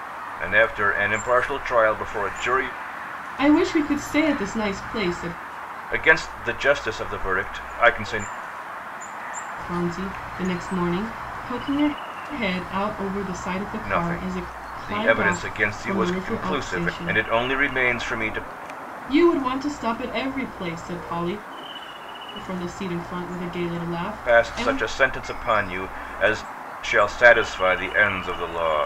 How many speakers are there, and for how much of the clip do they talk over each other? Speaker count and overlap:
two, about 13%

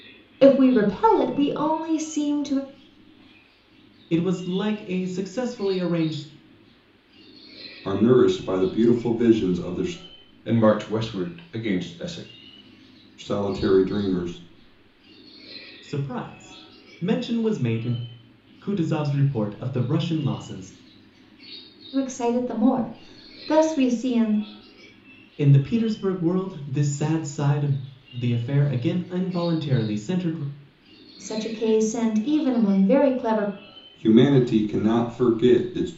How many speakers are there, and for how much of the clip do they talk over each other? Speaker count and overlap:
four, no overlap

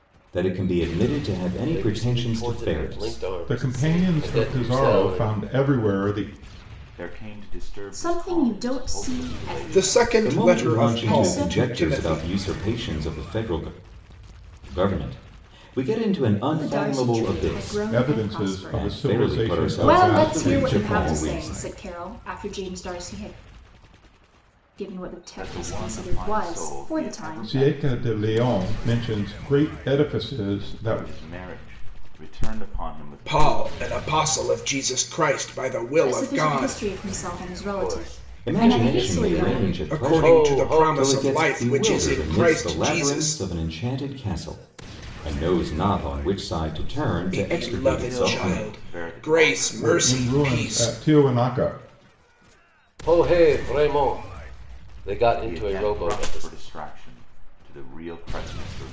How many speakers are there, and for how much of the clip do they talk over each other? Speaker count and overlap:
six, about 50%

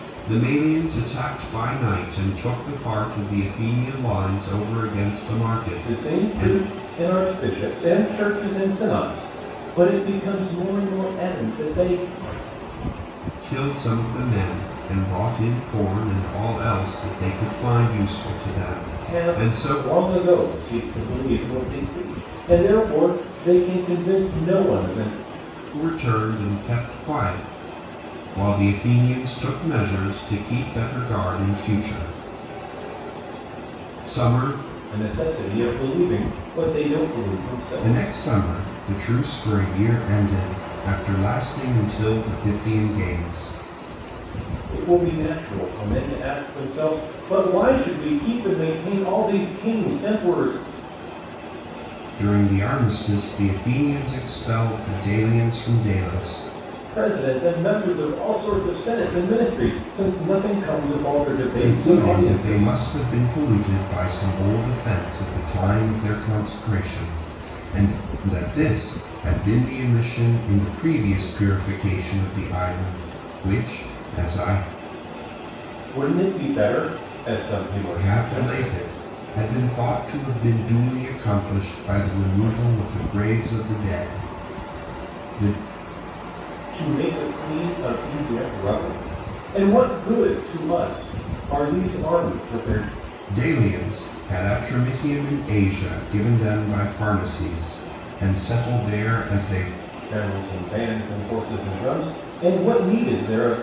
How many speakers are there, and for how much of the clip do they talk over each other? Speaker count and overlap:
two, about 4%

